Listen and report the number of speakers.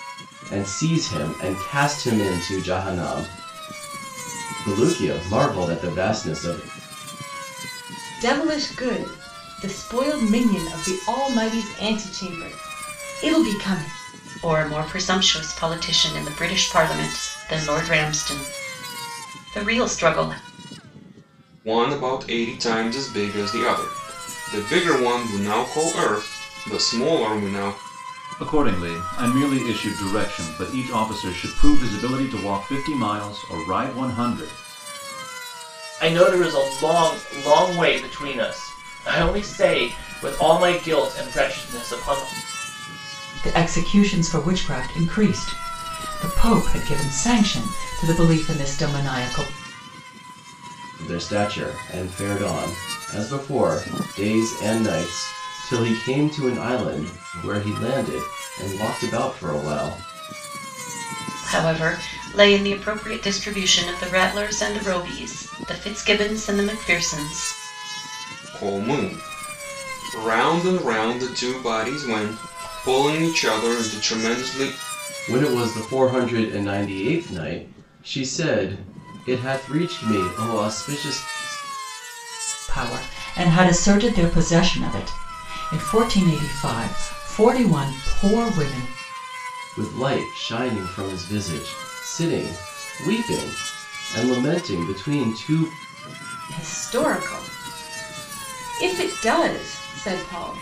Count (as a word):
seven